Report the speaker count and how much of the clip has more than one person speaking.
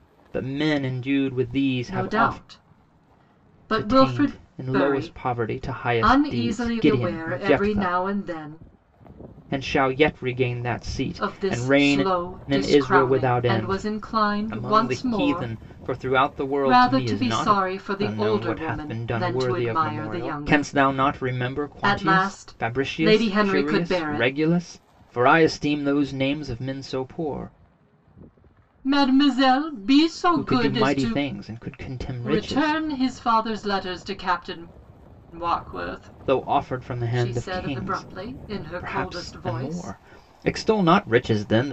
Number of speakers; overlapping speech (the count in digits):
2, about 46%